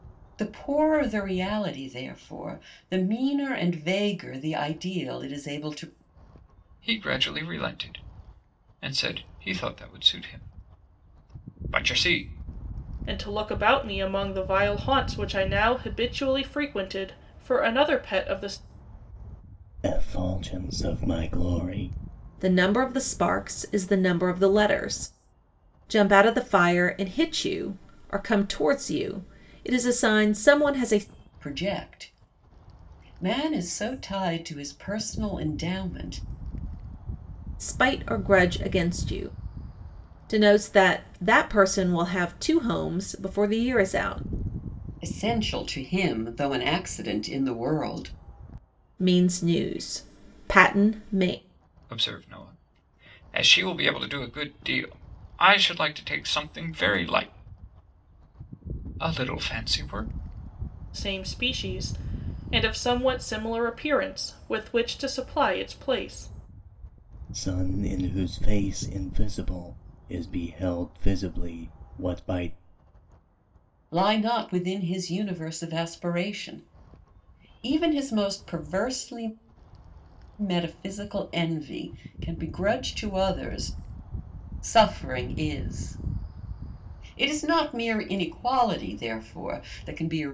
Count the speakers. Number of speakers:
five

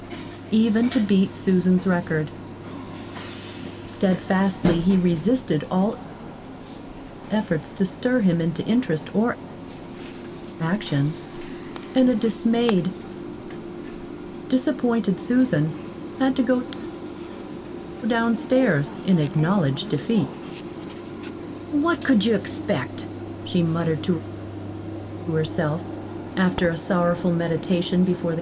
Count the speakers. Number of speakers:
one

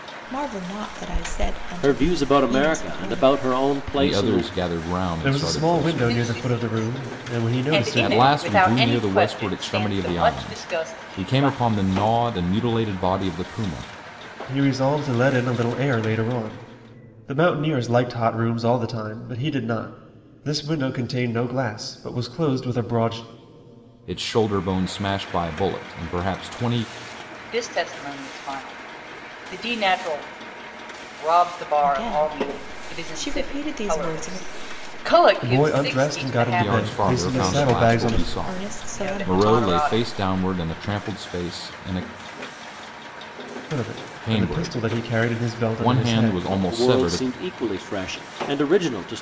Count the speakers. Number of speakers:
five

